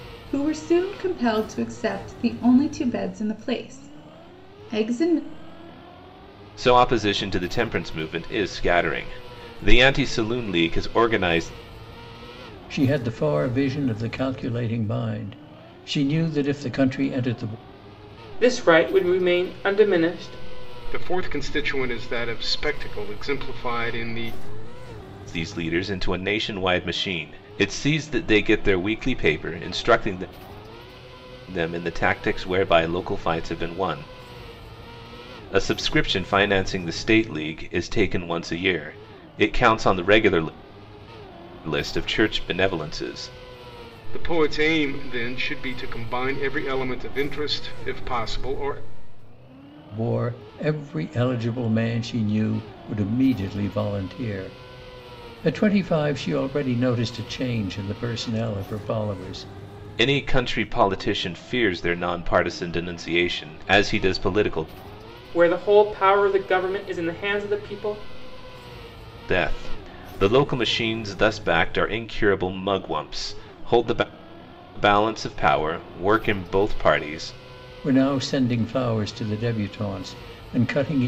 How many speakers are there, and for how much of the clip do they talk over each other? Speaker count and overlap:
five, no overlap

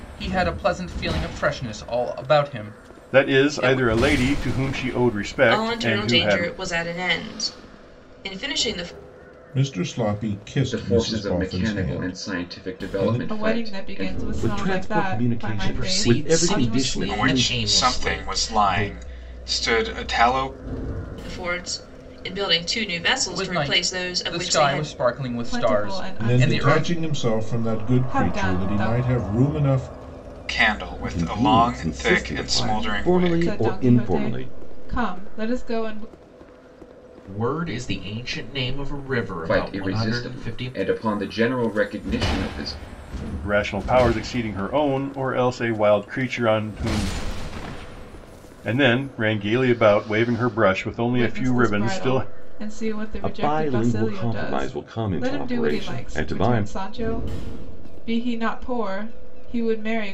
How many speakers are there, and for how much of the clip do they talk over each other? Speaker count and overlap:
nine, about 40%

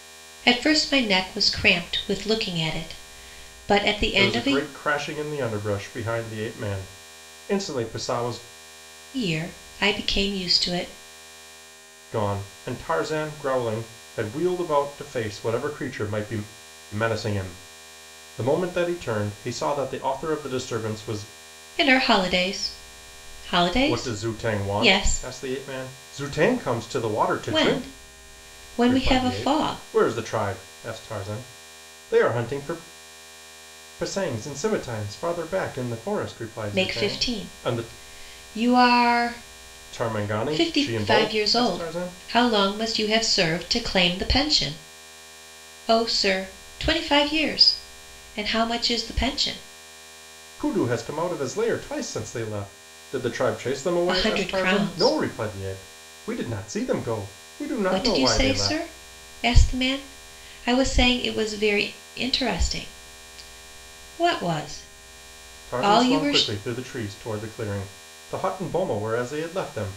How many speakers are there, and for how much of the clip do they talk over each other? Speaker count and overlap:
two, about 14%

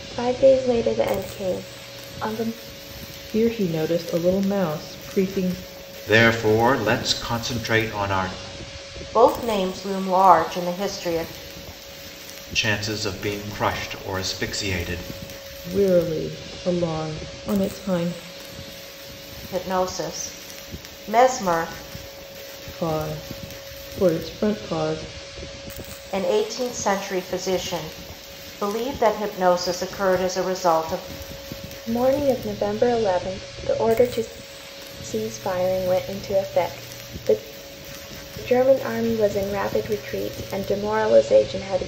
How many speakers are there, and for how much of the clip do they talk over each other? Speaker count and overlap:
four, no overlap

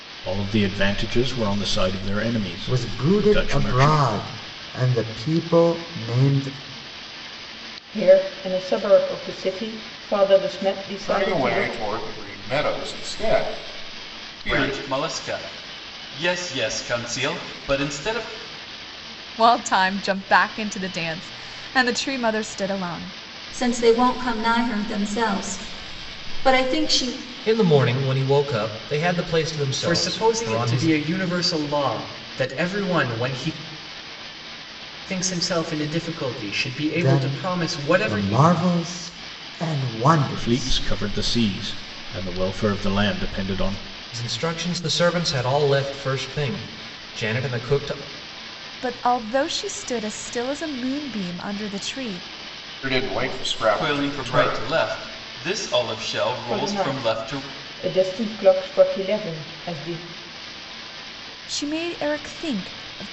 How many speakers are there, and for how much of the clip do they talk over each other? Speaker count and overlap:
nine, about 12%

